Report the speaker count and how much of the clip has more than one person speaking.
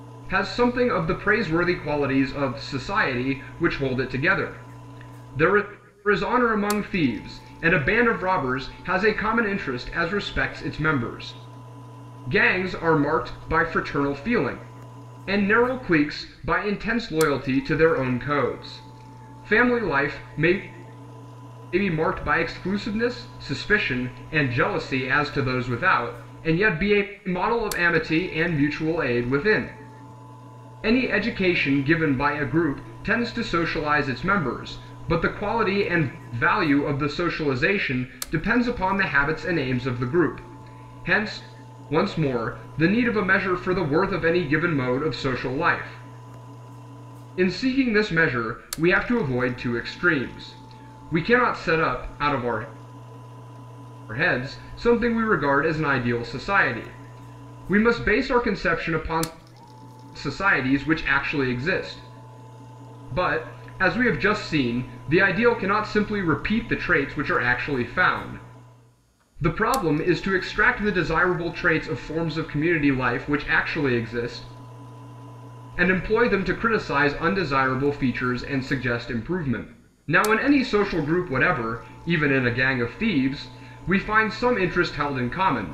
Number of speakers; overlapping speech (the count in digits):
1, no overlap